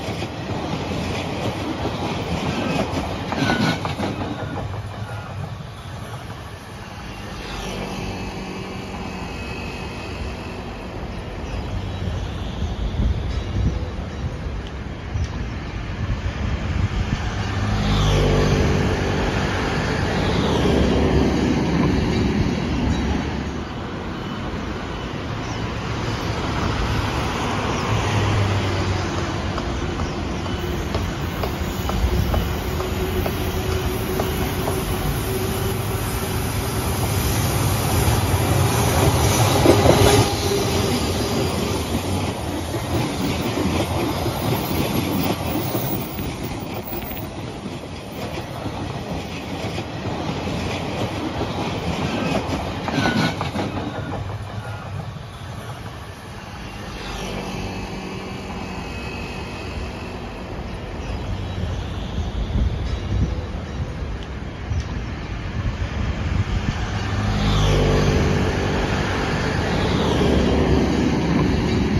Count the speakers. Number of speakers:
zero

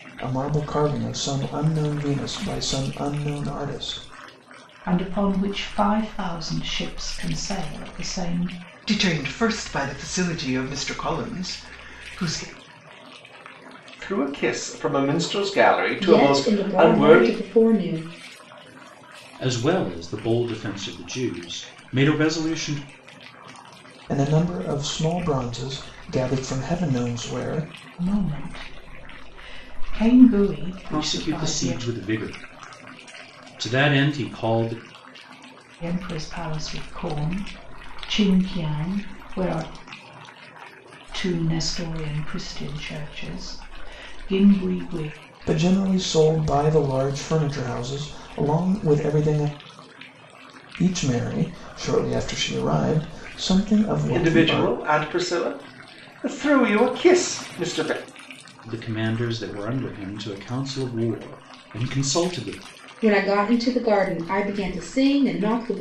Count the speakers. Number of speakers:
six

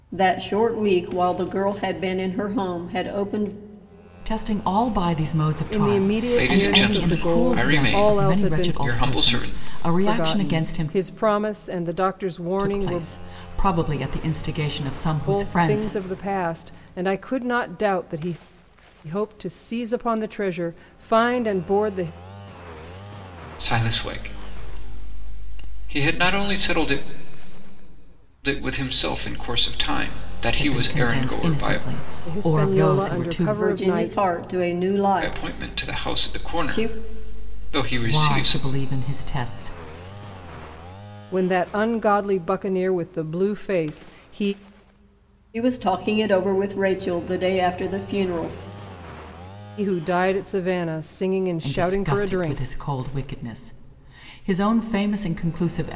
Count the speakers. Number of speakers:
four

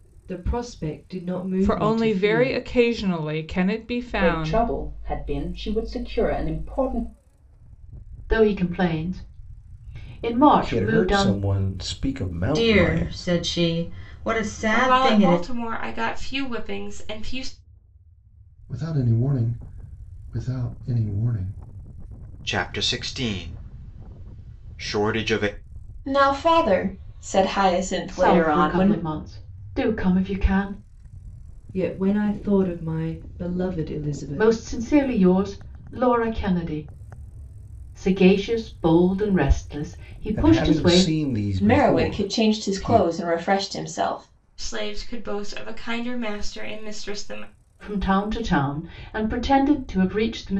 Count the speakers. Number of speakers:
ten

